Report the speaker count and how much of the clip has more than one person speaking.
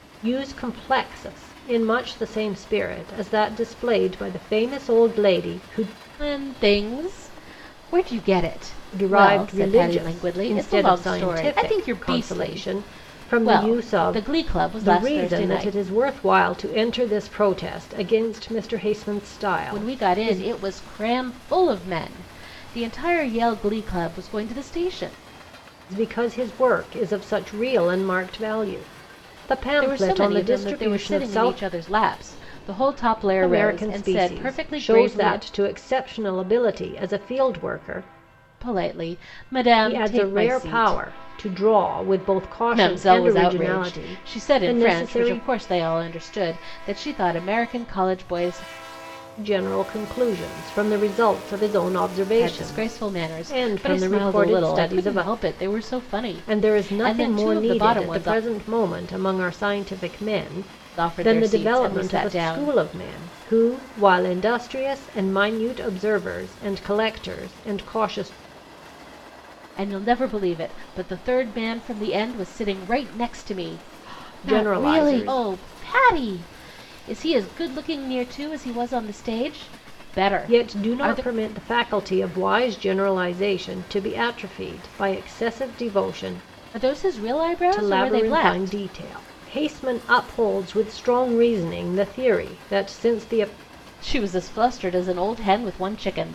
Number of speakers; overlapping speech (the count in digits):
2, about 26%